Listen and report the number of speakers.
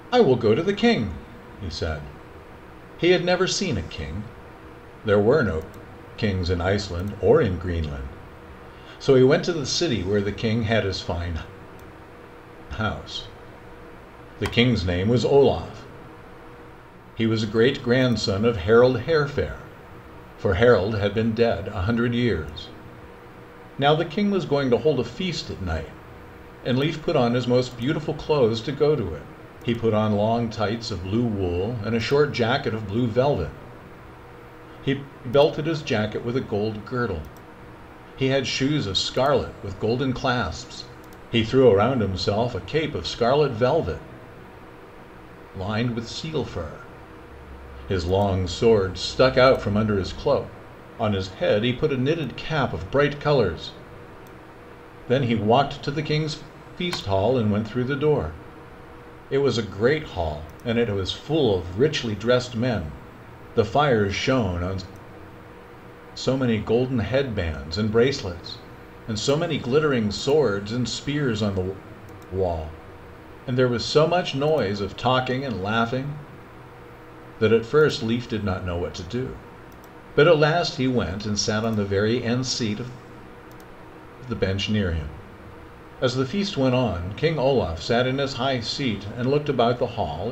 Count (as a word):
one